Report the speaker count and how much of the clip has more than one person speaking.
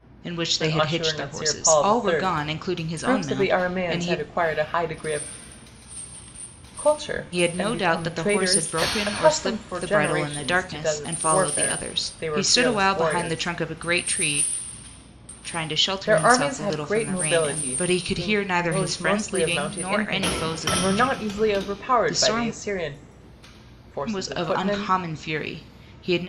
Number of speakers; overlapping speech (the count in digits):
2, about 62%